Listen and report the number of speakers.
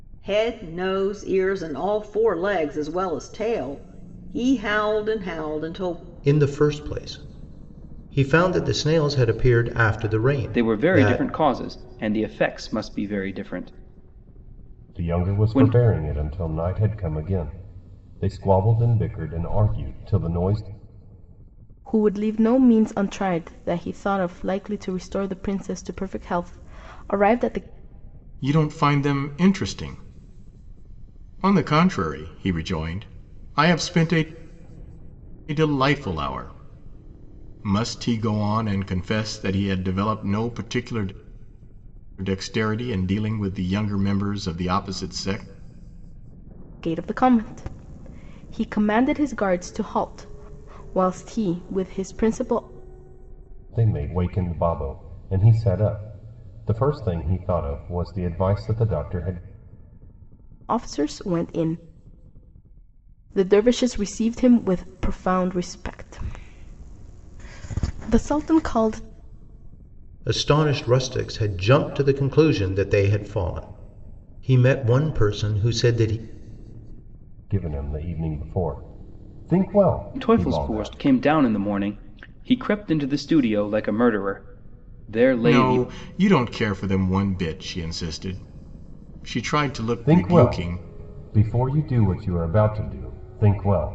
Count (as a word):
six